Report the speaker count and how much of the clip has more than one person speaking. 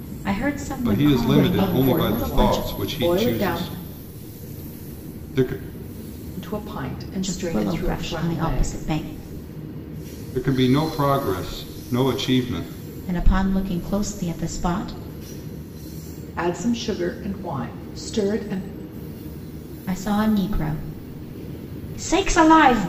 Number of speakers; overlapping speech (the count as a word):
three, about 20%